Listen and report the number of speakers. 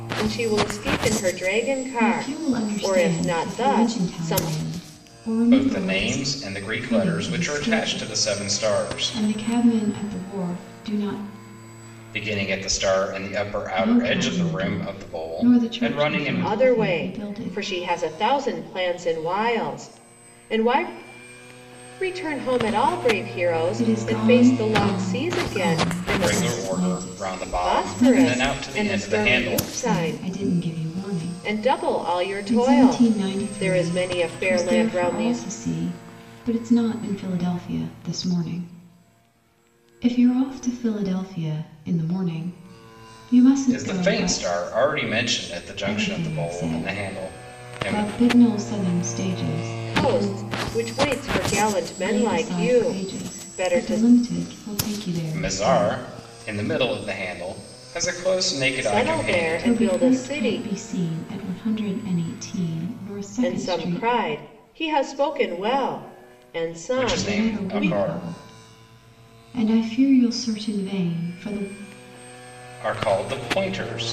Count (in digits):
3